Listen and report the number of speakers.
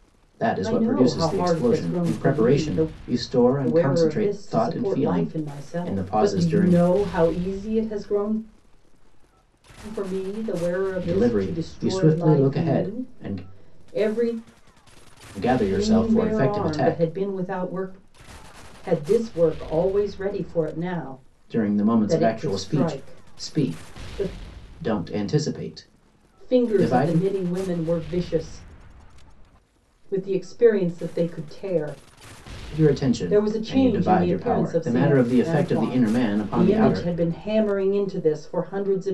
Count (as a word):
two